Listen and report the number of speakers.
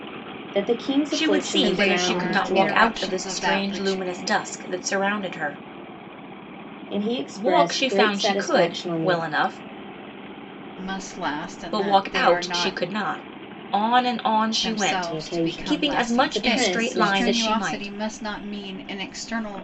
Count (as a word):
three